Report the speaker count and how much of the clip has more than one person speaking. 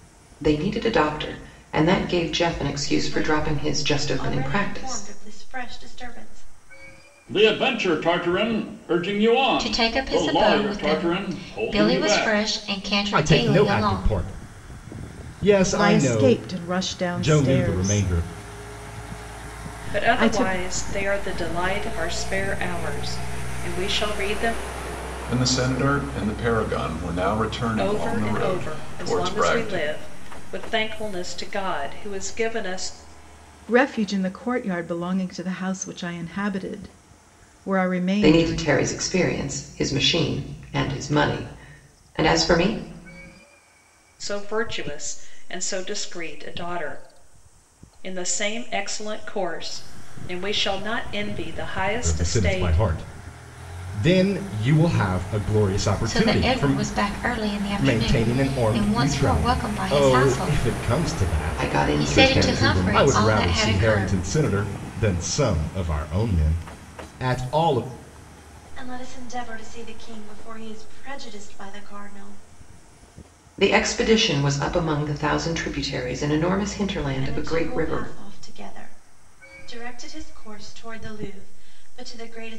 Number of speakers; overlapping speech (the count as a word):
eight, about 25%